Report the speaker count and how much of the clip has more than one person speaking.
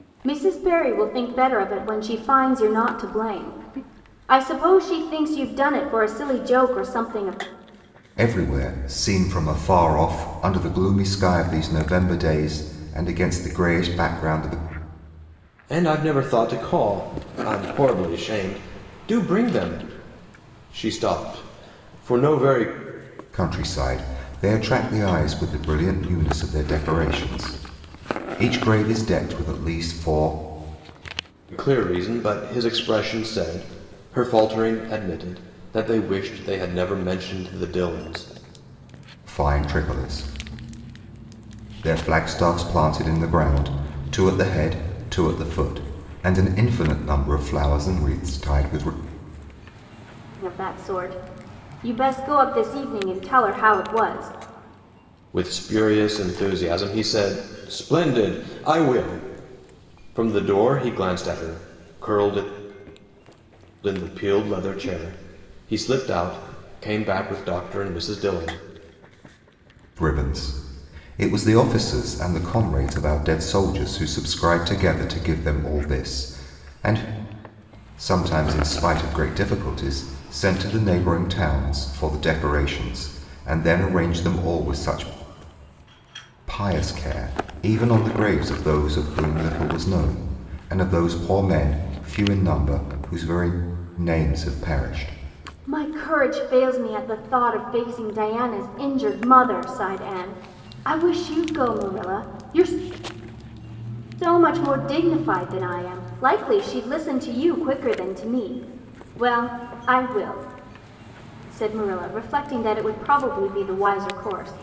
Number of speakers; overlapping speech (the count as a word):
three, no overlap